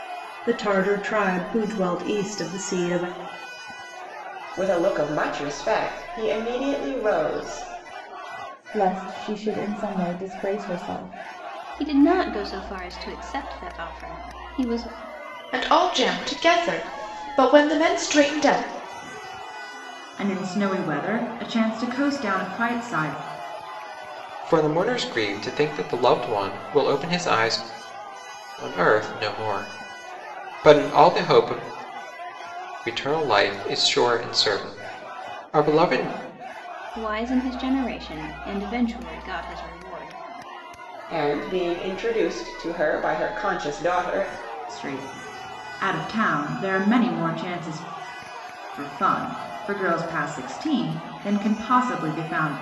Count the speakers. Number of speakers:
7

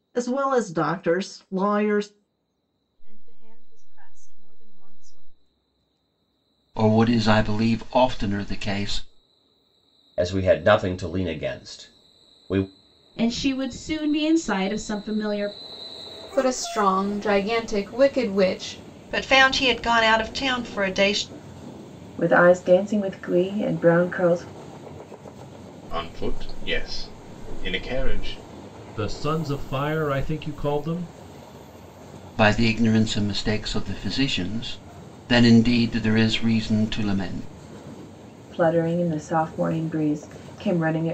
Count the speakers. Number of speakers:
10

